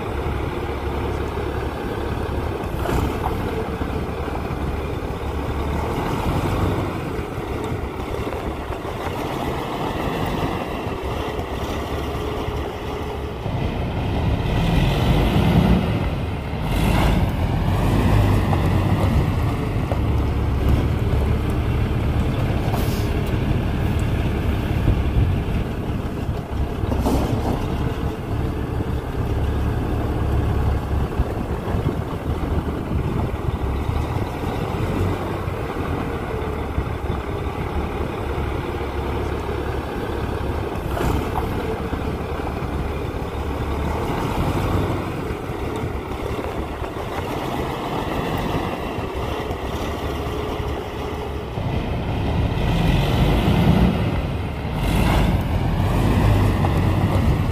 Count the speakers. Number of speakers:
zero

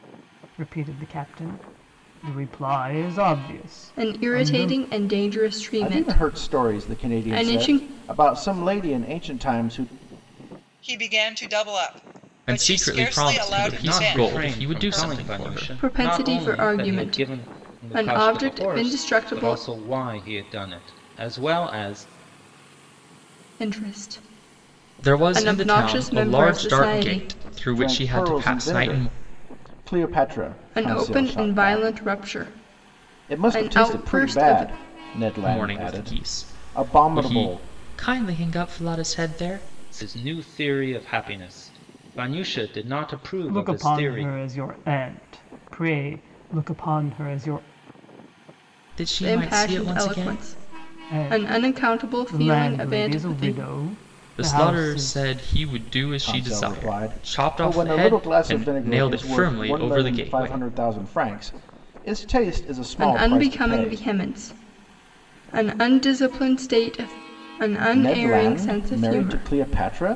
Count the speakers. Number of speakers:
six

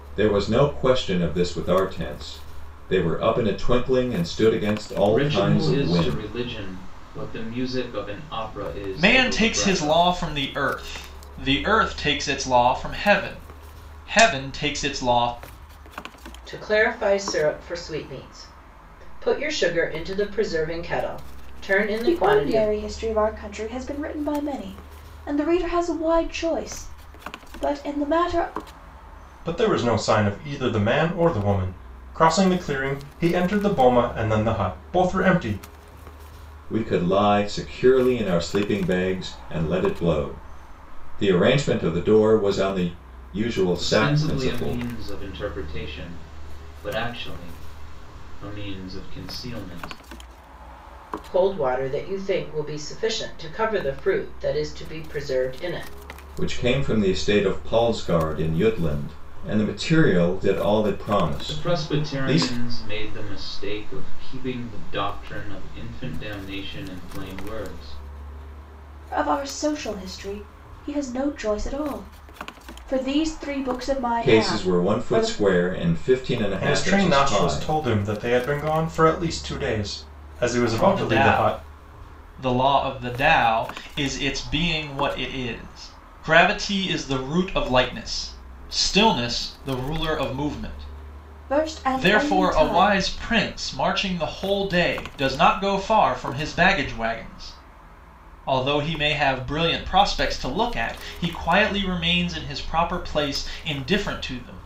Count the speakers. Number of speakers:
six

